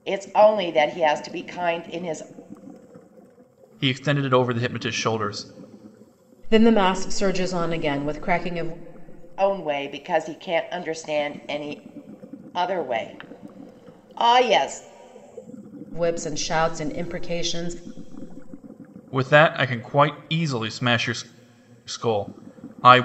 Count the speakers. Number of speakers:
3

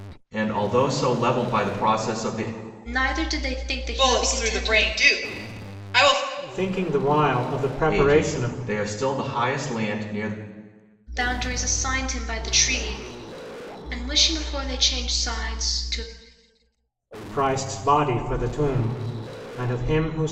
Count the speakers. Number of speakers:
4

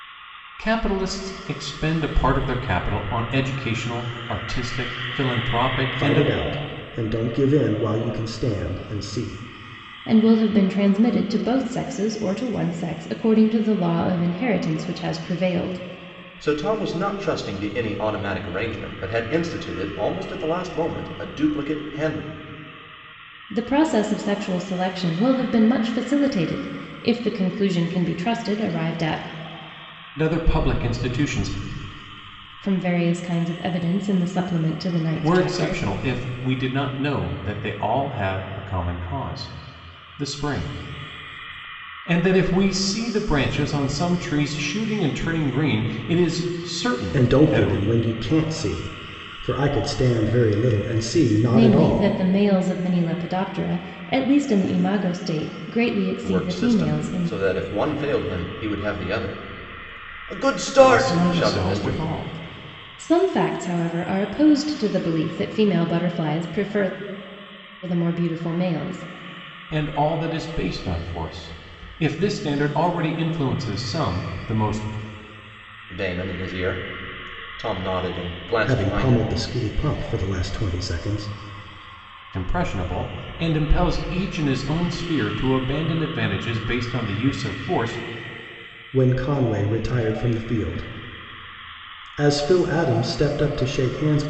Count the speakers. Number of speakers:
4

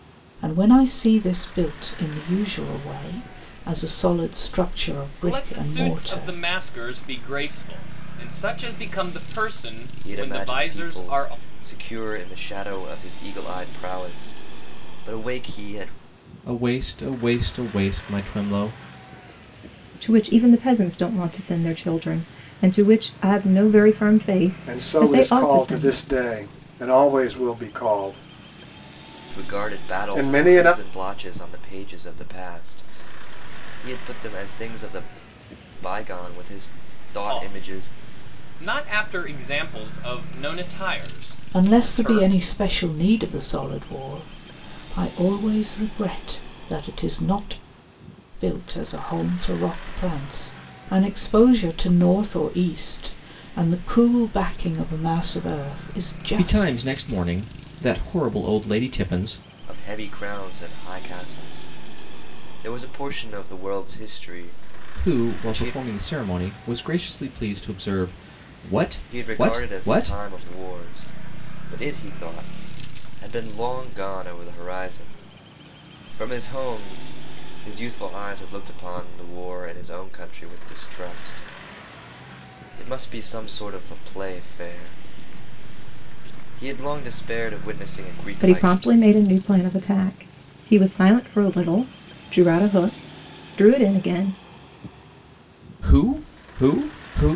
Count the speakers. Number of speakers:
6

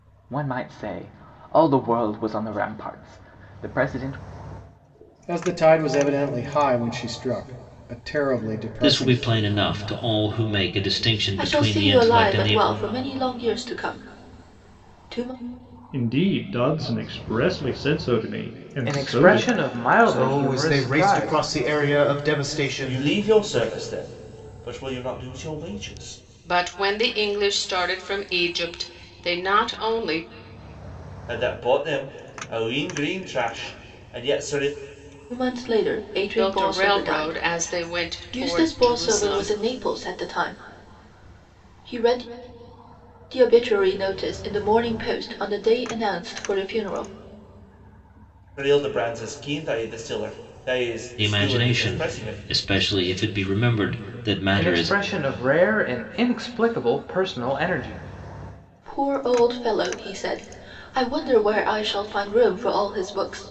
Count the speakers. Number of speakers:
9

